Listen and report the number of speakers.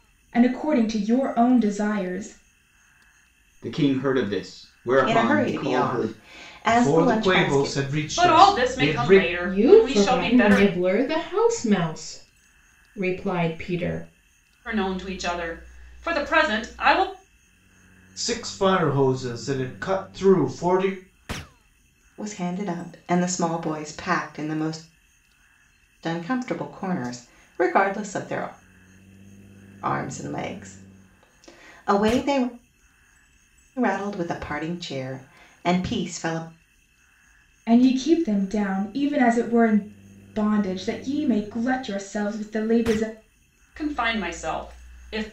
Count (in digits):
6